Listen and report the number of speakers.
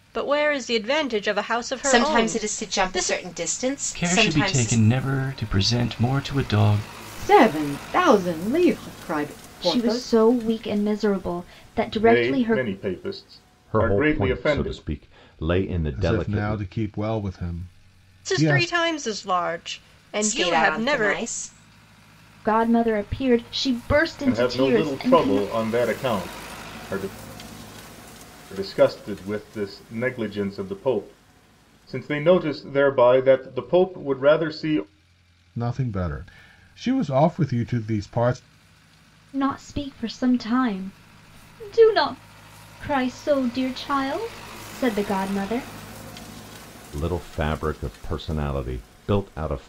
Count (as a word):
eight